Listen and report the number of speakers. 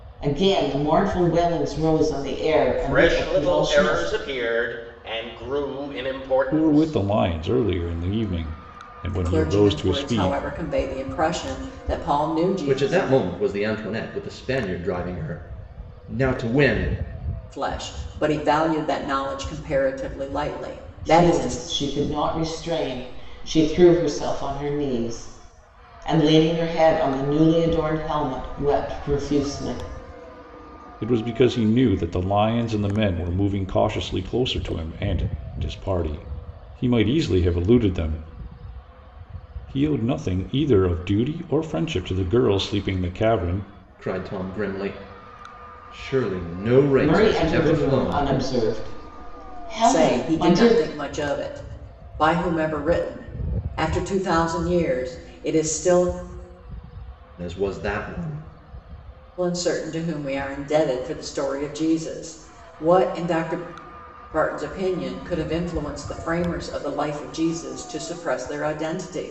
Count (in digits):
5